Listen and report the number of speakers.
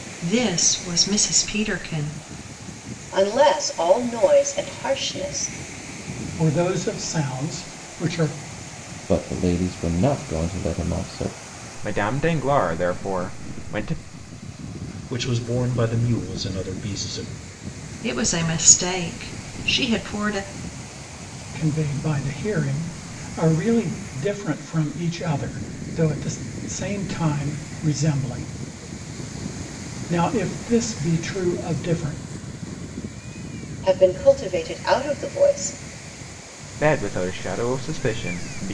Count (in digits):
6